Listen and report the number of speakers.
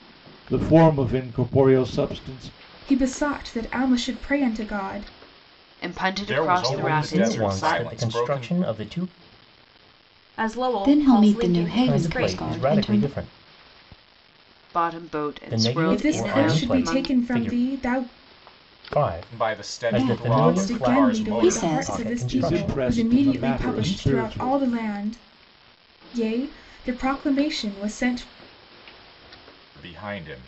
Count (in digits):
7